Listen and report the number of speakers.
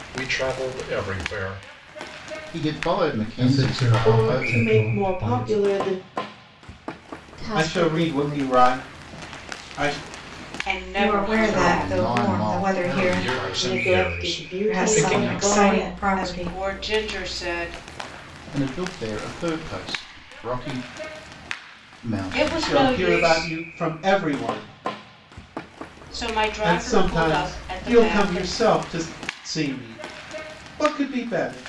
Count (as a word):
eight